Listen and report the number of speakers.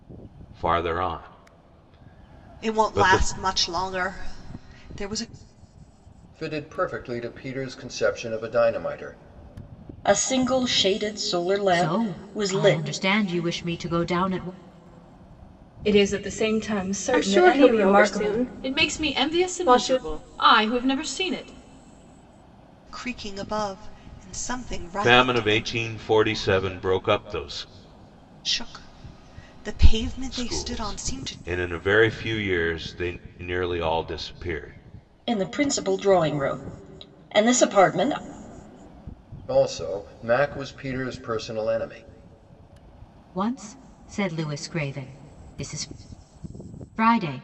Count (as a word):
eight